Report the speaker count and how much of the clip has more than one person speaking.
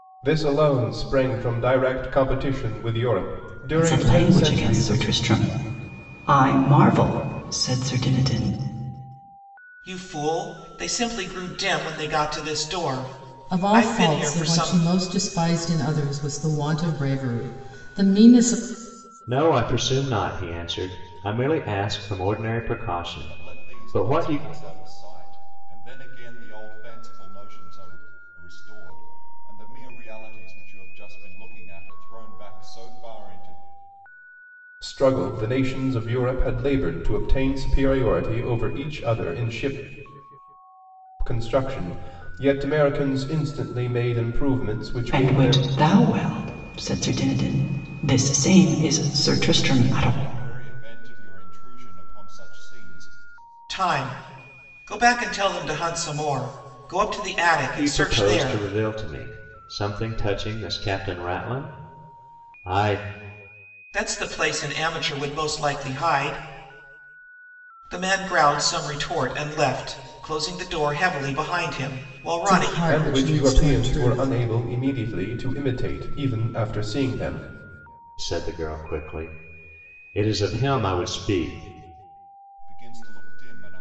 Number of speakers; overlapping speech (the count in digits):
6, about 10%